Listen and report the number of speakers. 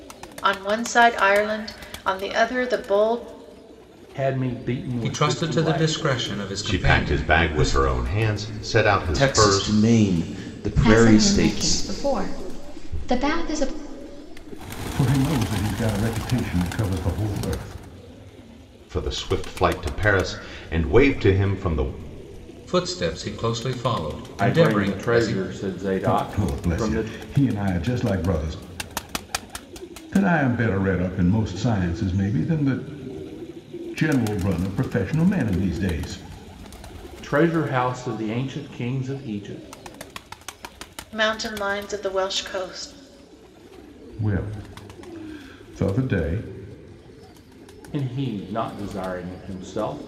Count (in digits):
7